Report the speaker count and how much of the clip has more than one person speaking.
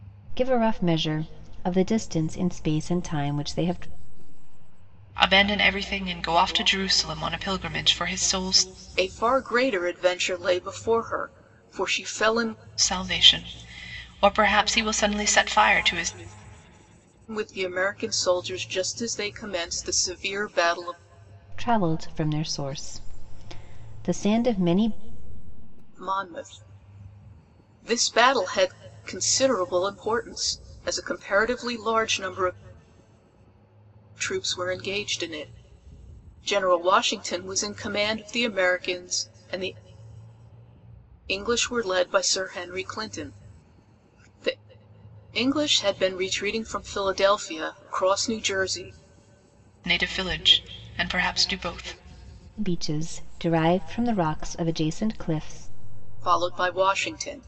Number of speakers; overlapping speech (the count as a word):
three, no overlap